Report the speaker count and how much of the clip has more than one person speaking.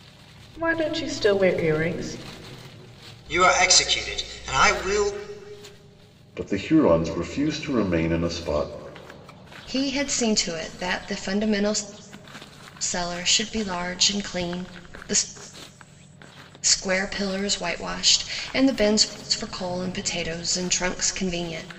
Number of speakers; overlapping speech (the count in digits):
4, no overlap